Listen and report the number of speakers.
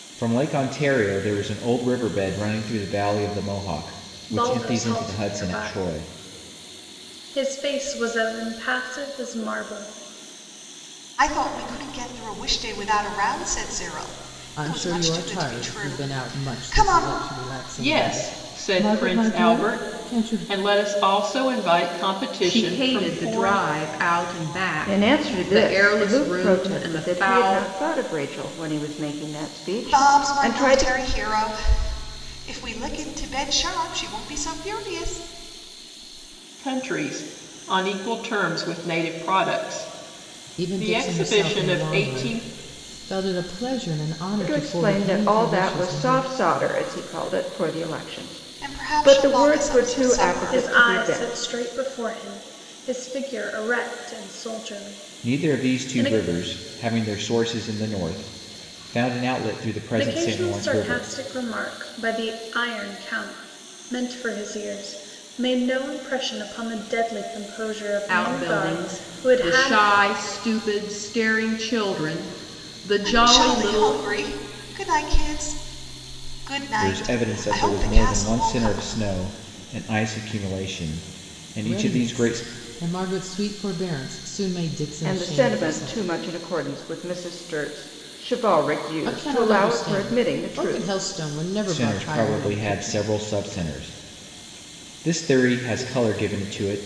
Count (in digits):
7